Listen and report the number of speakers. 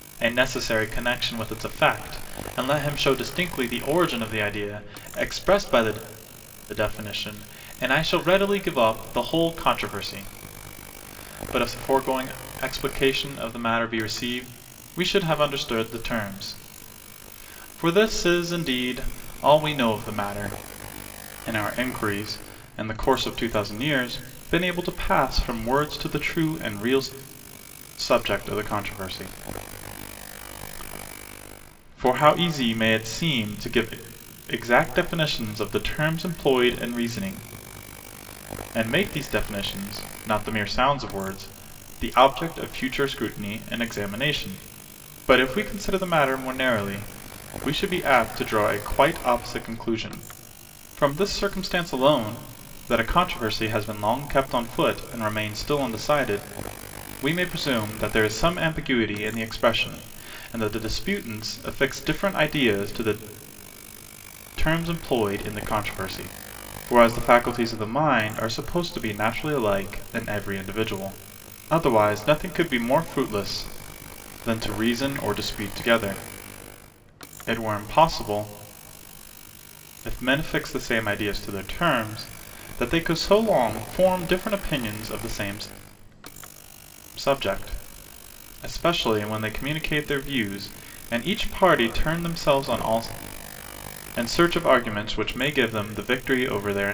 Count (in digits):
1